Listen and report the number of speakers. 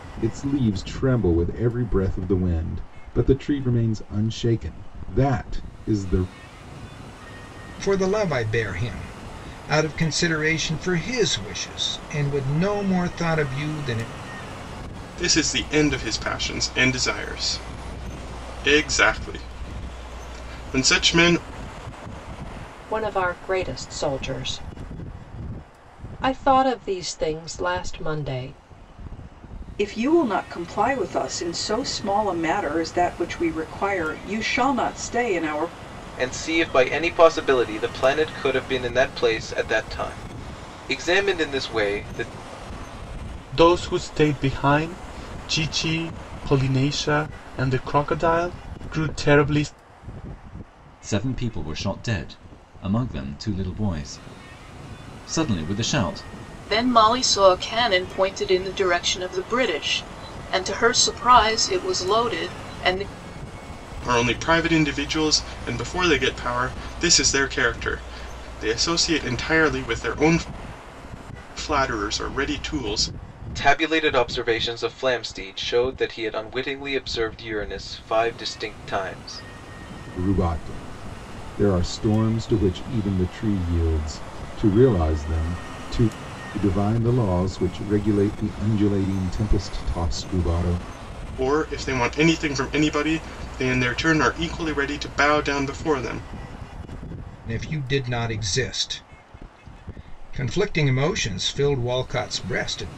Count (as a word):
nine